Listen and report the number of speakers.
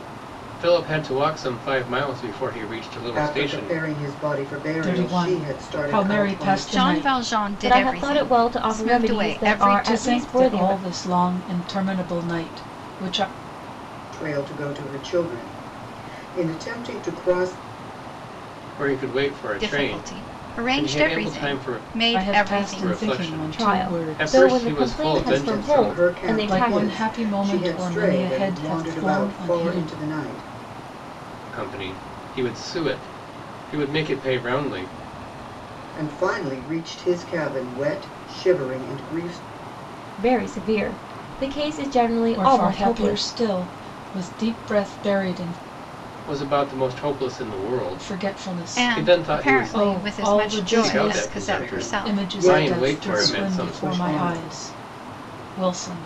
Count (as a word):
five